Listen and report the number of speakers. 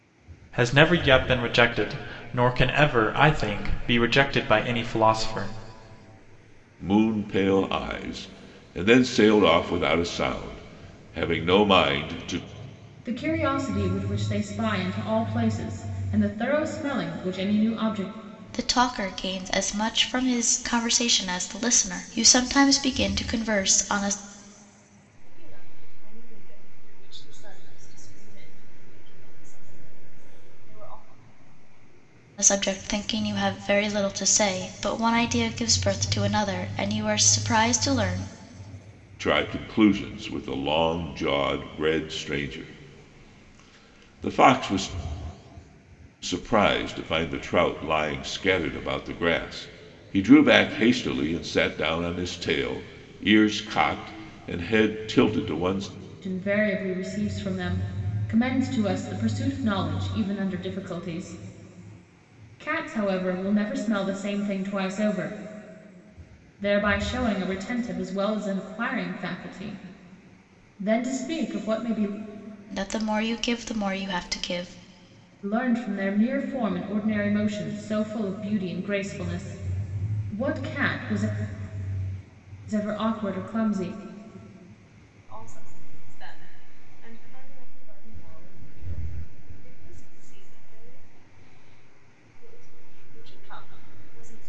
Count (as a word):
five